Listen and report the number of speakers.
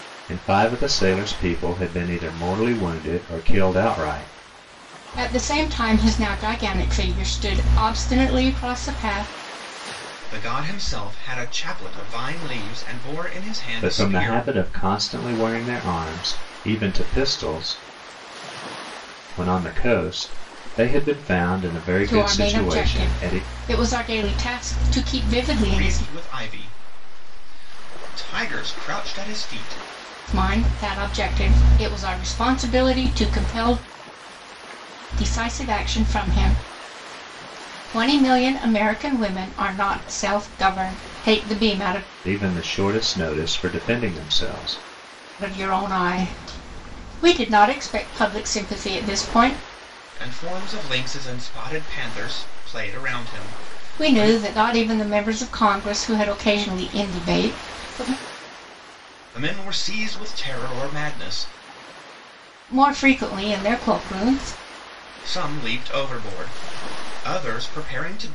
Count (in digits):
3